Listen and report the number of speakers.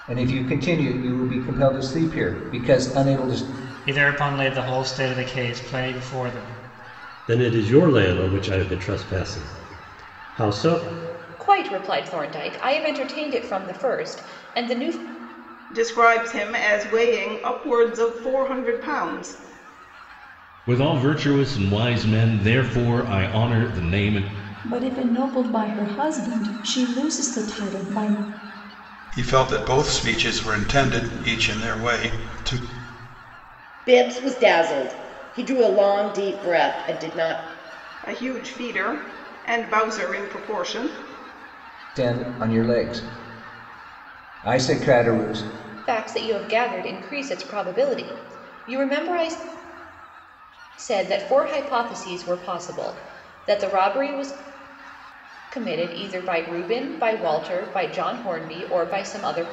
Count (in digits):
9